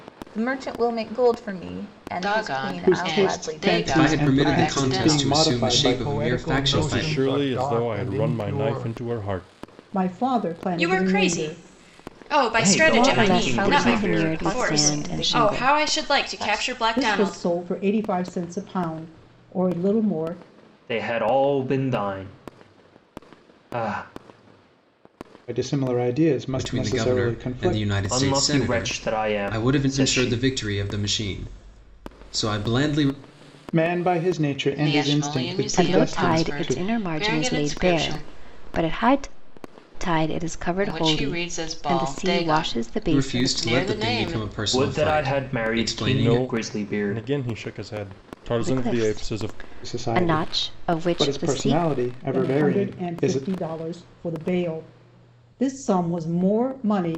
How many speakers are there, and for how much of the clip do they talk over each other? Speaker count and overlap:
ten, about 53%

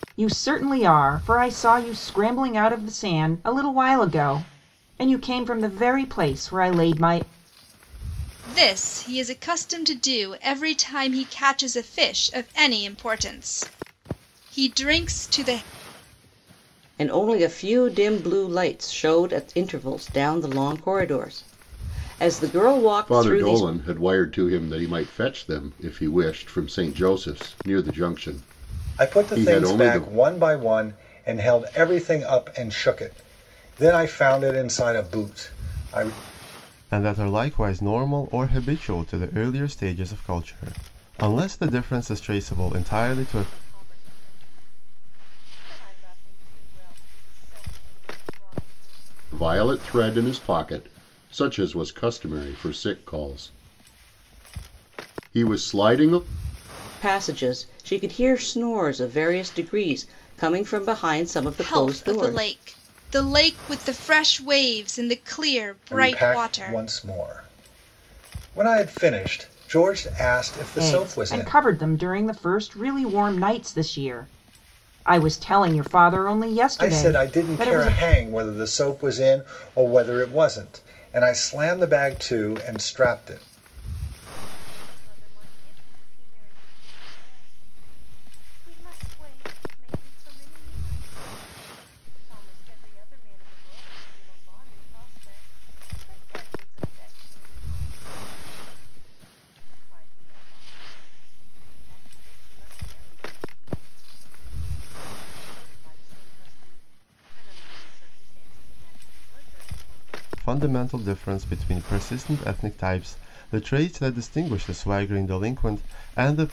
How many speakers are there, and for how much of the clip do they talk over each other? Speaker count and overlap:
seven, about 7%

